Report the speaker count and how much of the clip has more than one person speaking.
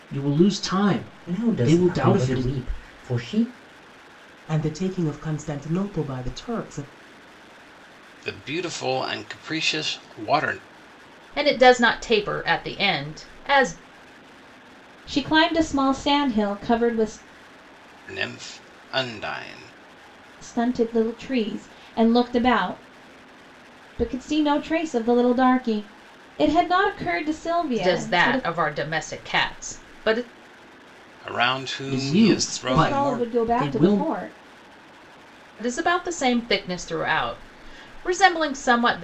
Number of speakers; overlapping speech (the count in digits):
6, about 10%